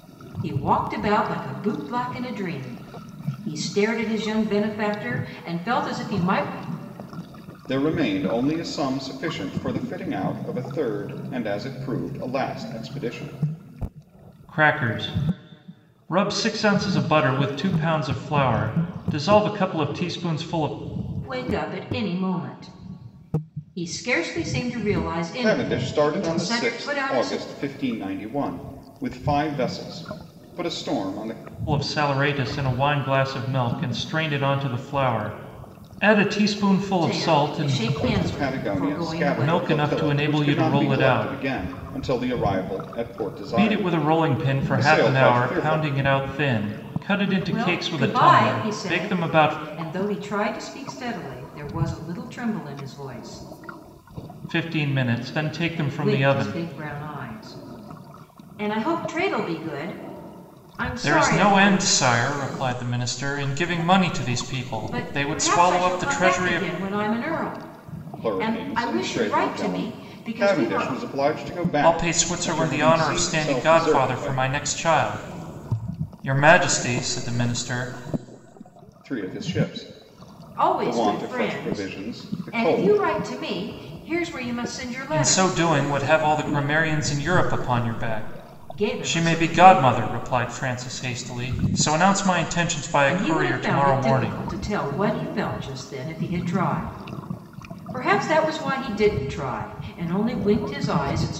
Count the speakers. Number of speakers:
three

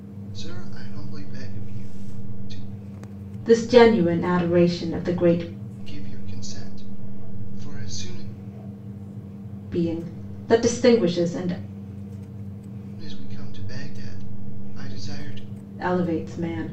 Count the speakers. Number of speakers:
two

